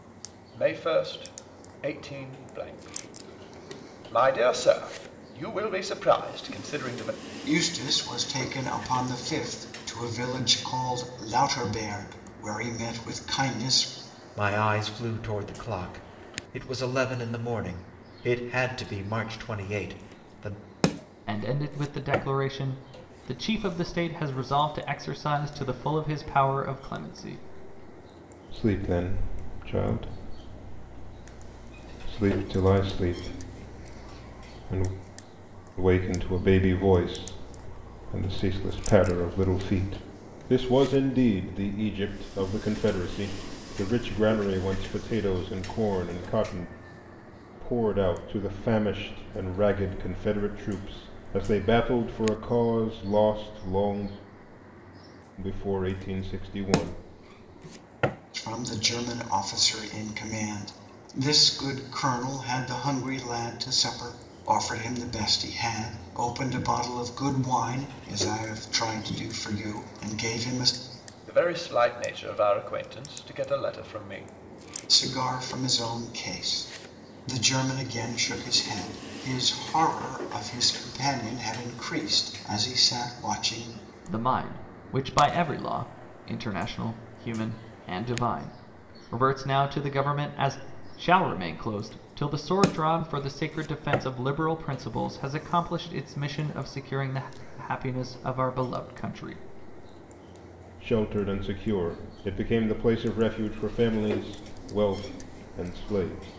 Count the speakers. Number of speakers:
five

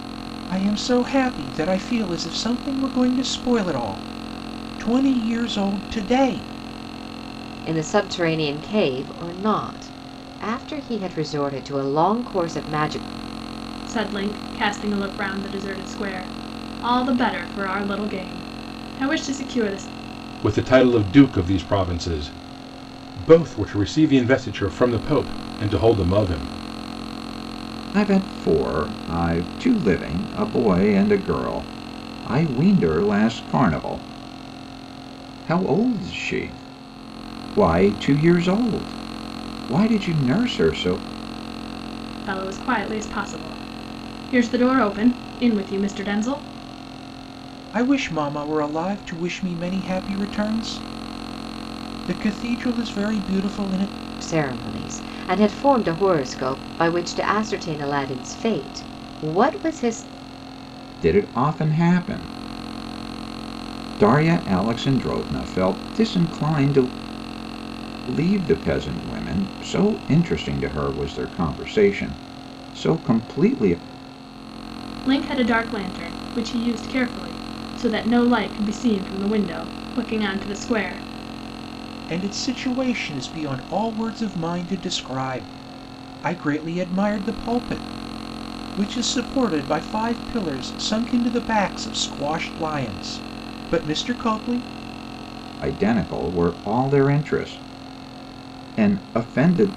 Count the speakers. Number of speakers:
five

